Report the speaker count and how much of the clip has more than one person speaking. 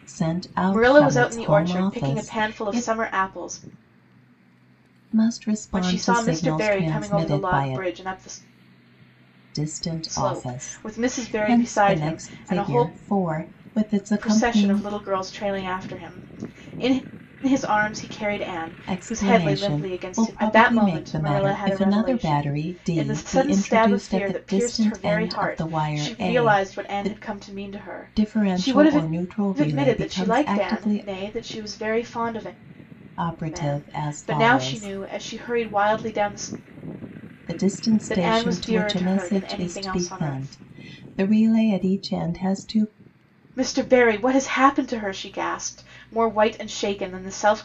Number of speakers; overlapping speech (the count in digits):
2, about 48%